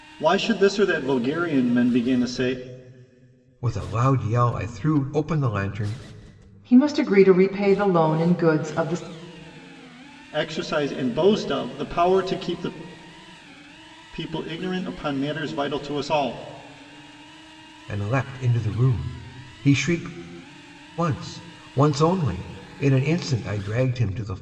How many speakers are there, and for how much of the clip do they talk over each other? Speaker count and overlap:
three, no overlap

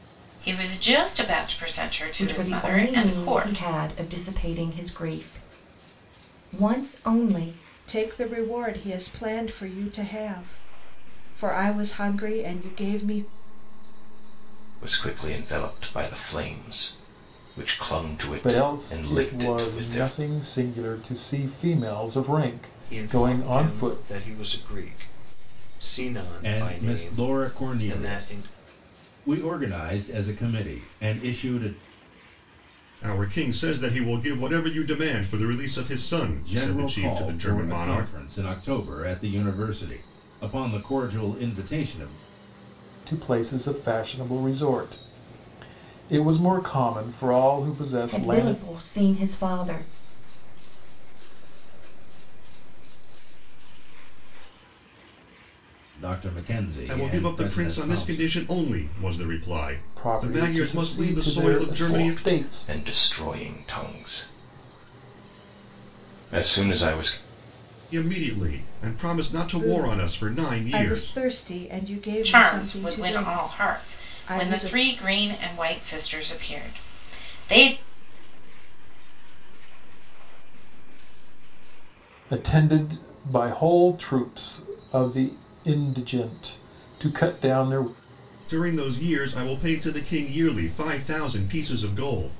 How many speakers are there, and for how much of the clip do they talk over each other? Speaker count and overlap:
nine, about 27%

